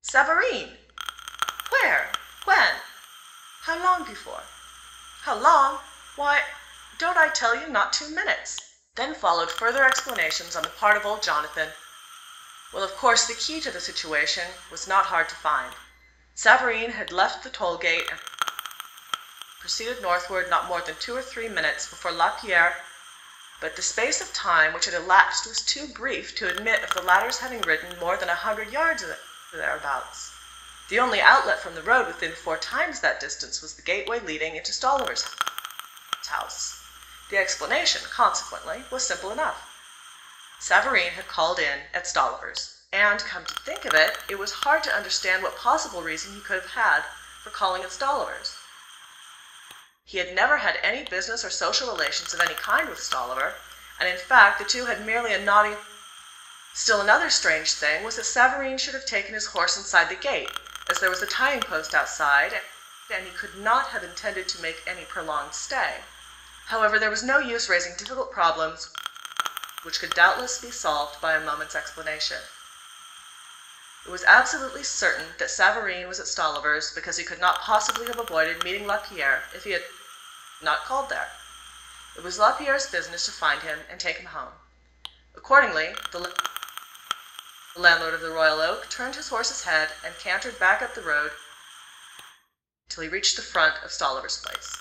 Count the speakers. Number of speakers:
1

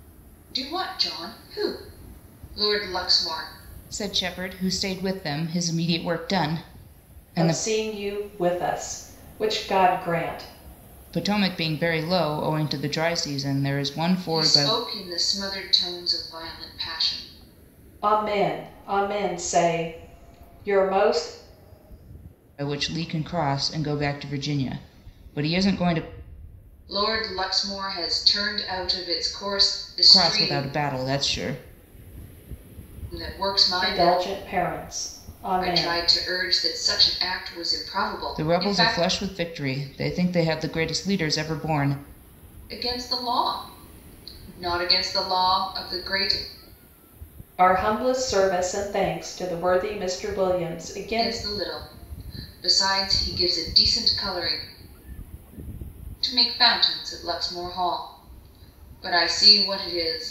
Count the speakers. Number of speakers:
3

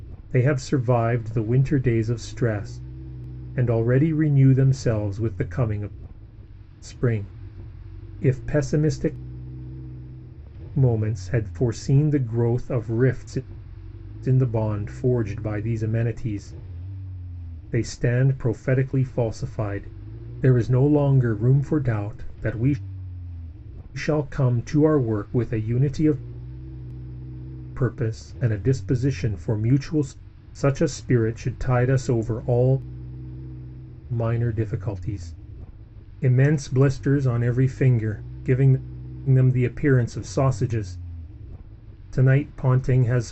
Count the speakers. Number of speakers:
1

